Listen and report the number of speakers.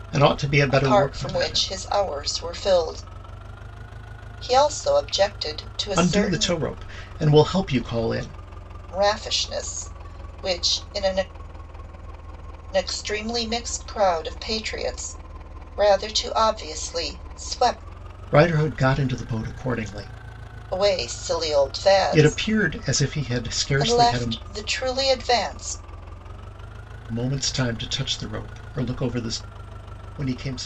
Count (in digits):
2